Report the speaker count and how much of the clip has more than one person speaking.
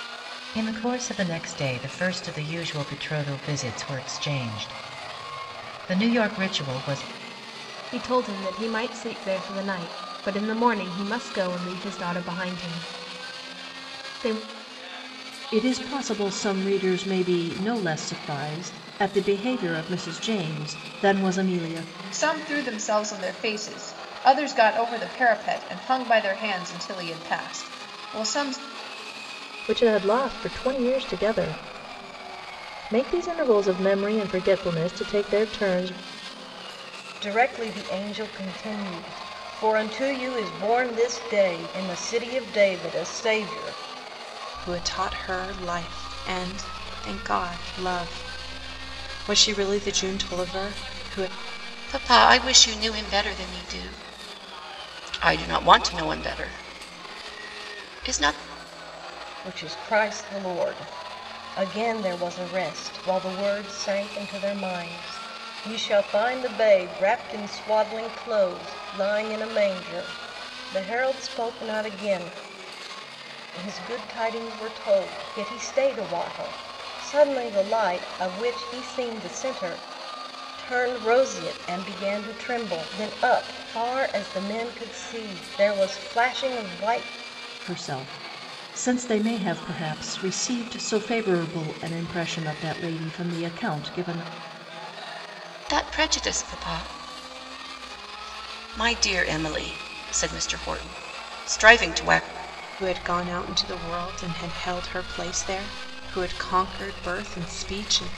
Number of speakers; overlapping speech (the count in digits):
8, no overlap